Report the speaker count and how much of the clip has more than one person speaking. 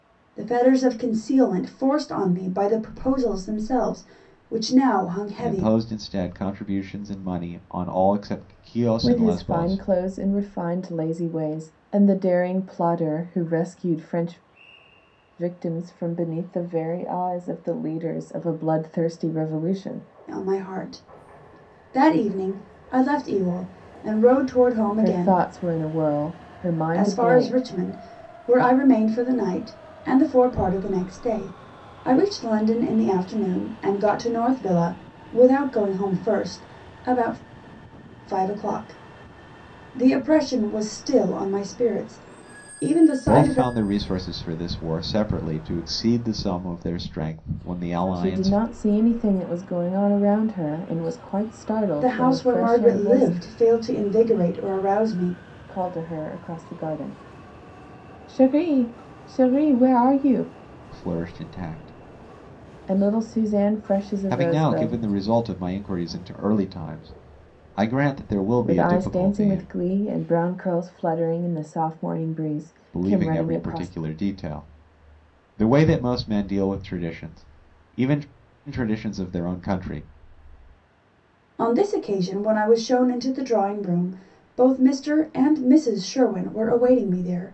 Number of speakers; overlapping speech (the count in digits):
3, about 9%